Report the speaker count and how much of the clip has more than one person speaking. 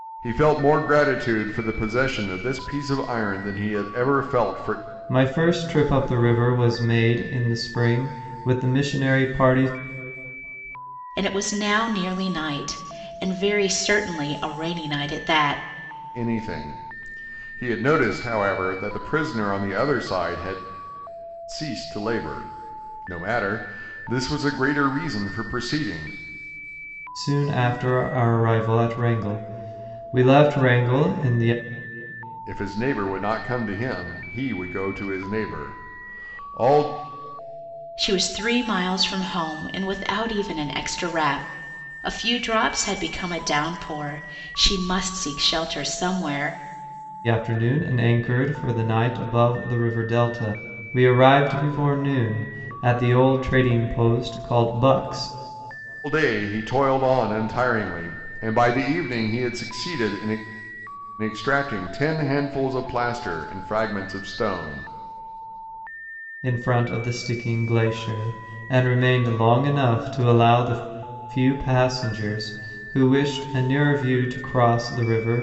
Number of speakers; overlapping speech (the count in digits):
3, no overlap